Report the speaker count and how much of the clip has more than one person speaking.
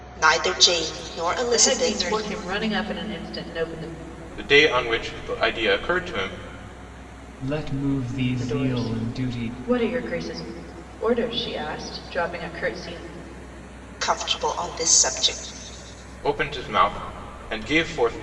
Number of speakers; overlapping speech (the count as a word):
four, about 11%